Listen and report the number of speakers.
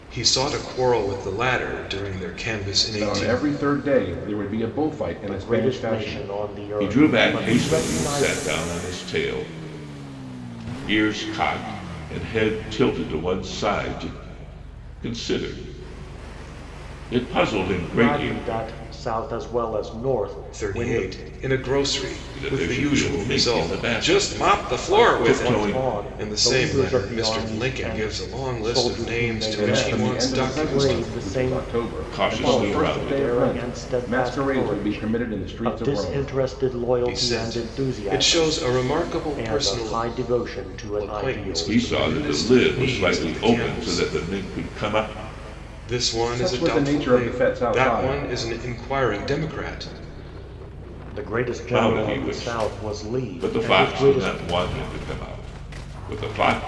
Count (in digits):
4